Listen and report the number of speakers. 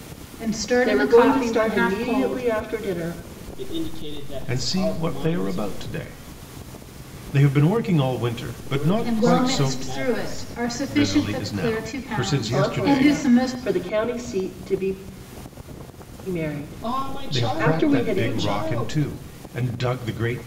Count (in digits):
4